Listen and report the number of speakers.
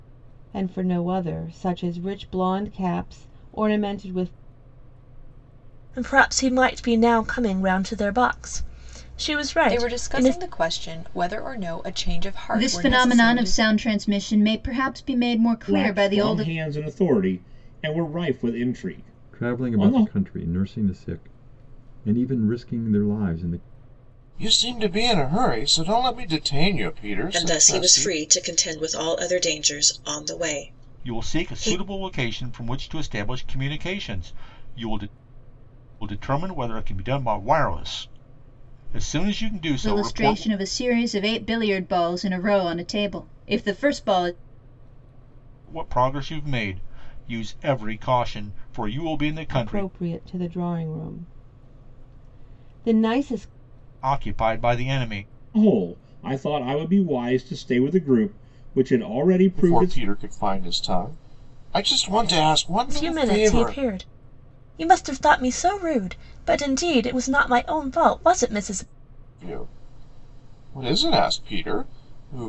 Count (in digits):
9